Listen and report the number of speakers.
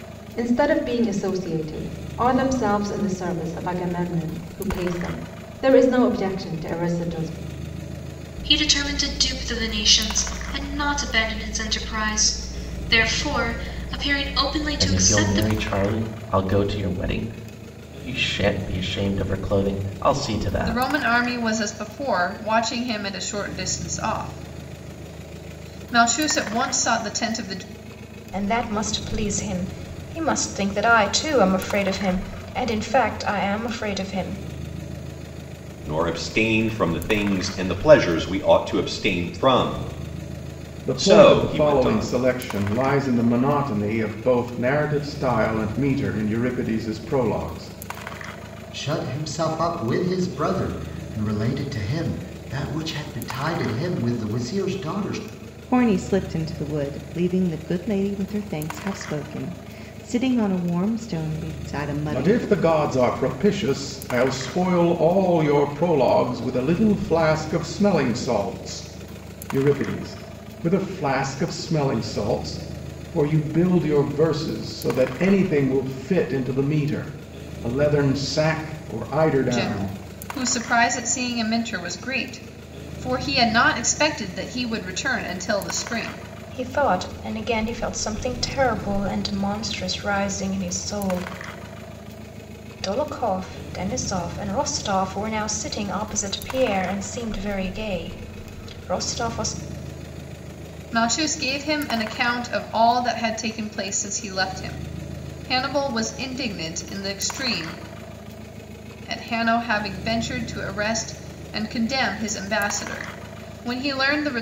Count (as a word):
nine